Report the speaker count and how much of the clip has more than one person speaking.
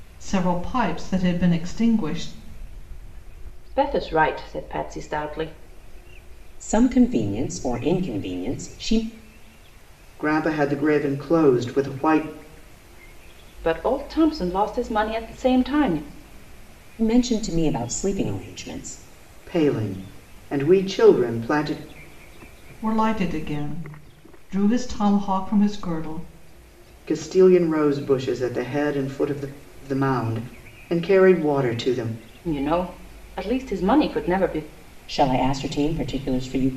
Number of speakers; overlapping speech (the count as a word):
four, no overlap